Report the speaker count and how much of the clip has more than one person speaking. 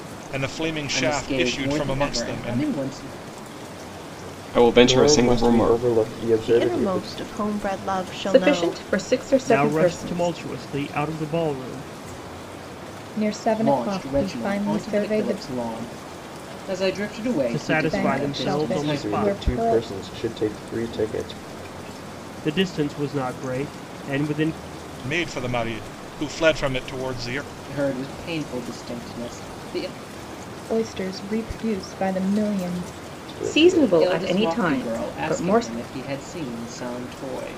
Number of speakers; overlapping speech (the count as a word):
eight, about 31%